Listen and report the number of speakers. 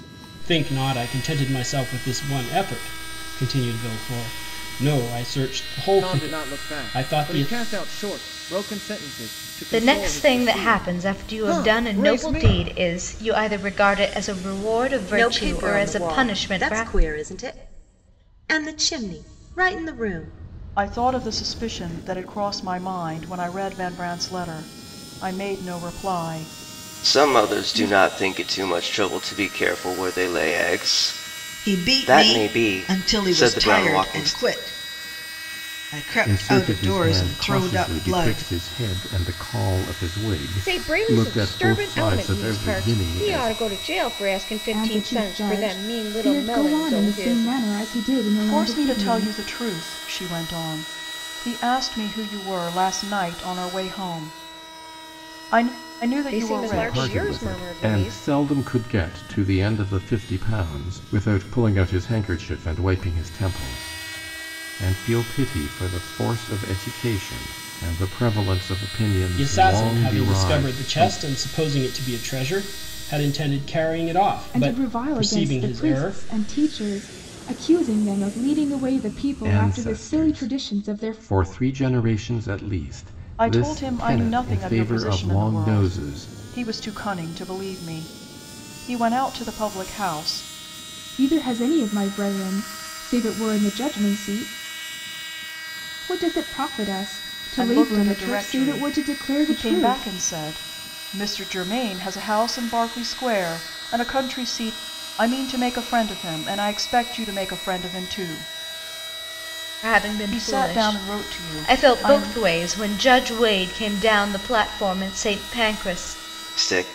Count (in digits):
10